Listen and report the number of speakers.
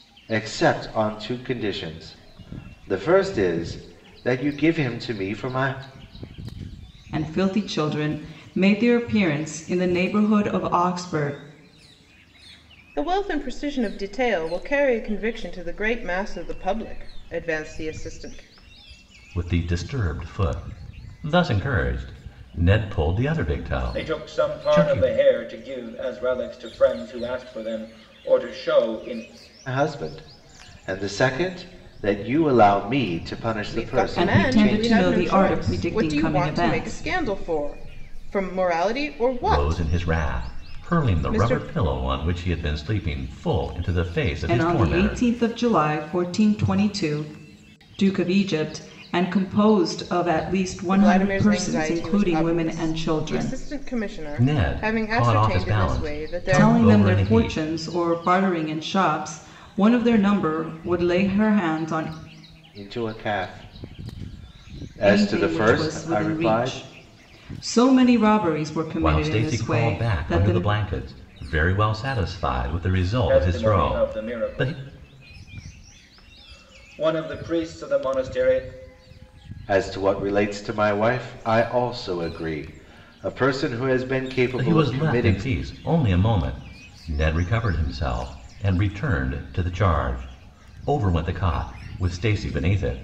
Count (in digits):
5